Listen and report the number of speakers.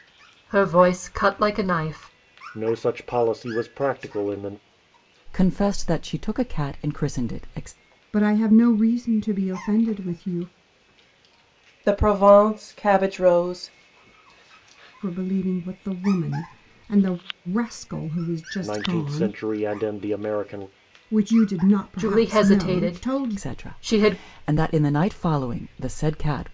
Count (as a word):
five